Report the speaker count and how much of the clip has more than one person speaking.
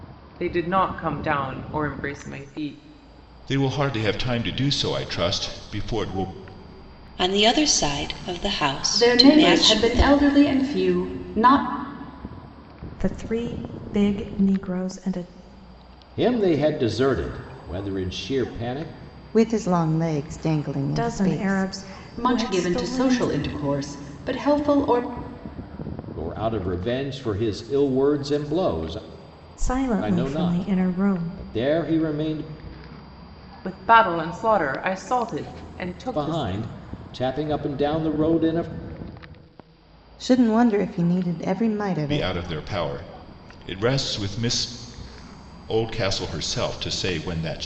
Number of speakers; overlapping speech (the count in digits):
7, about 11%